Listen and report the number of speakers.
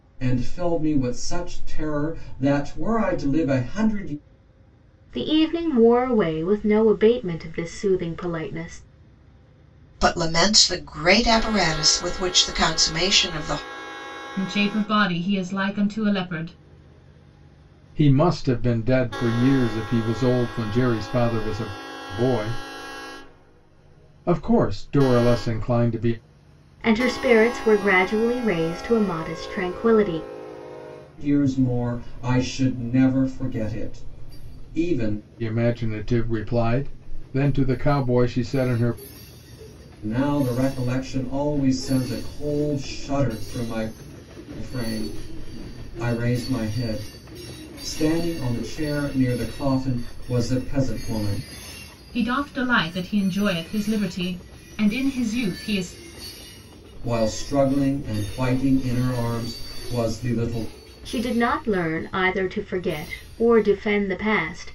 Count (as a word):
five